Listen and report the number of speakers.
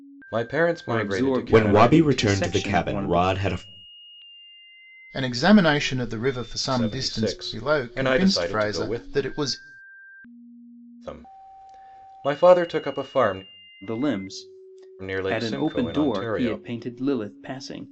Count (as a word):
four